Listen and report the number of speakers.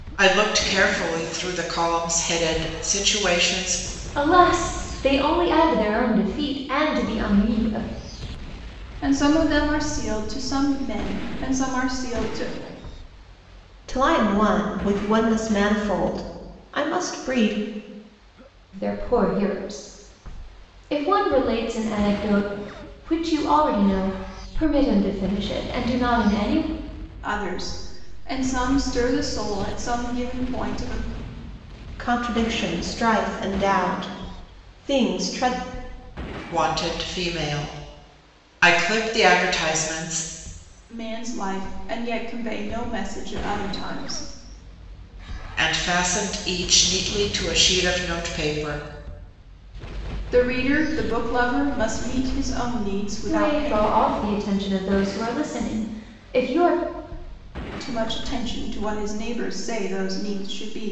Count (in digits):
4